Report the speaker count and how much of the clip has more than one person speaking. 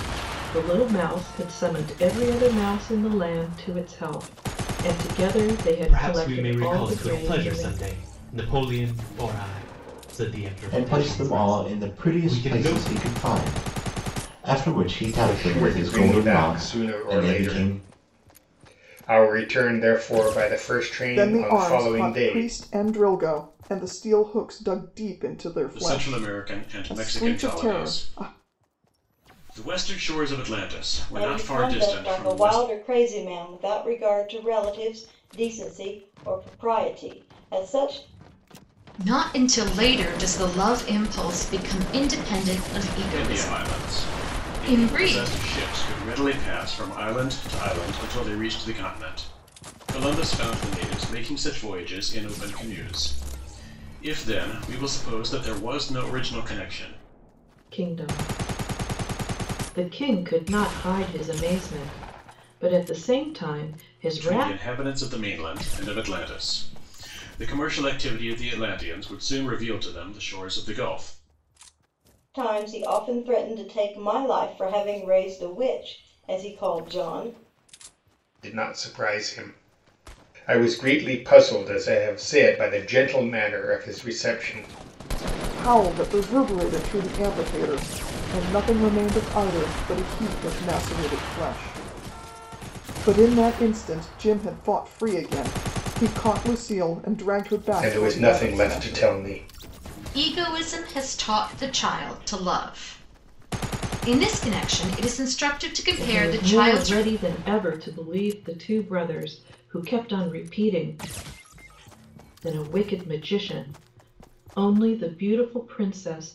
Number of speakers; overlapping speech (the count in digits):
8, about 15%